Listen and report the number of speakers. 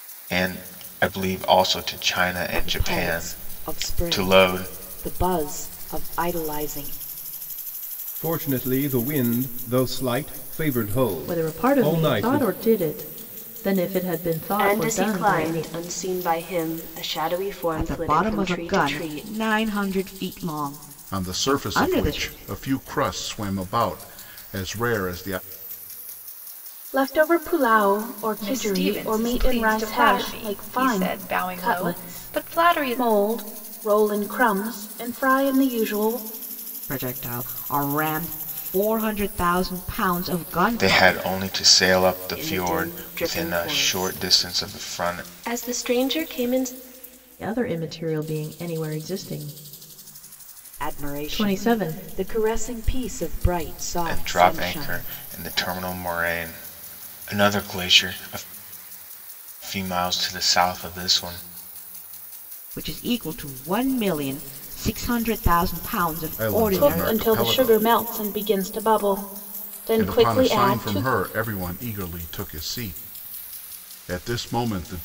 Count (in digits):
9